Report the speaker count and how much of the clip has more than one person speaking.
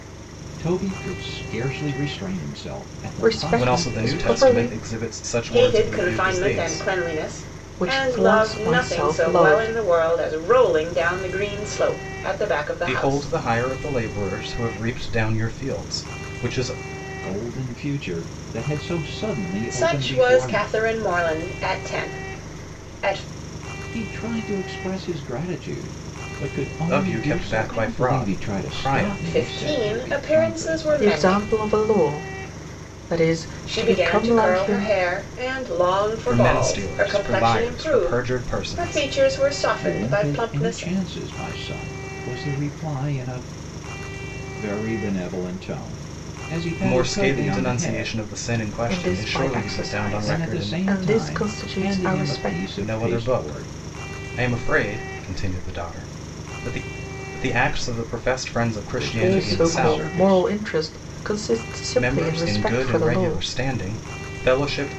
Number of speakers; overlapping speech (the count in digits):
4, about 40%